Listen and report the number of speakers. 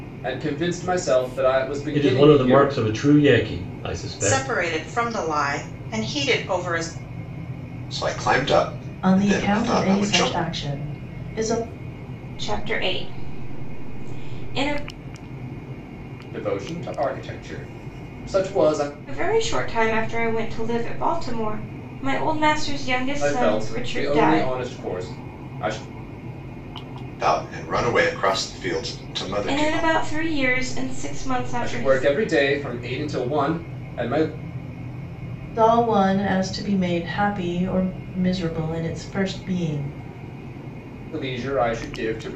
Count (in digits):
6